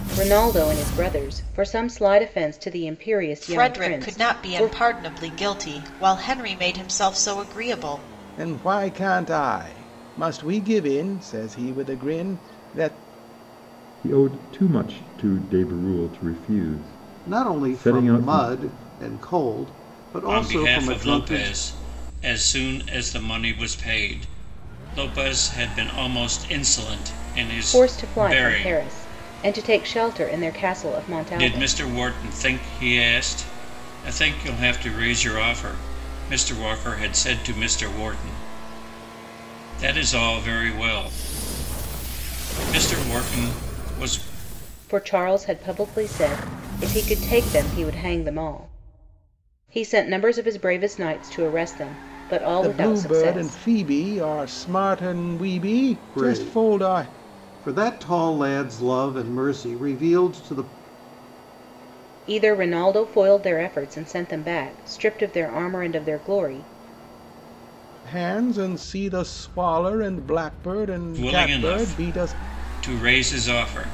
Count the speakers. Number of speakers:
6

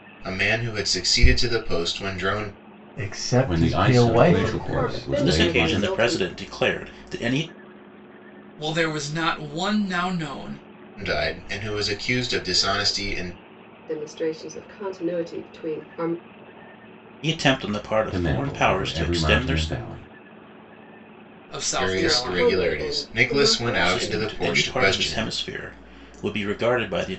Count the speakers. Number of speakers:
6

